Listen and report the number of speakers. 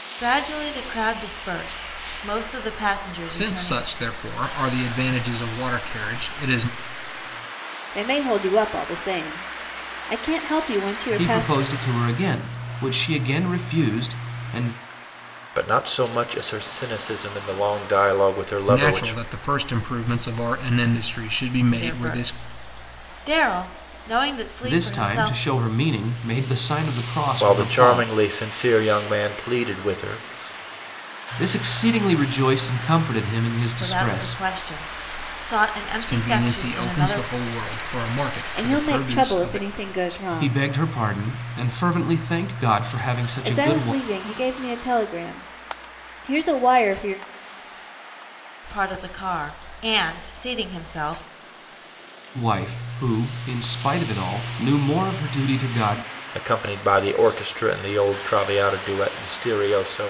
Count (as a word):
five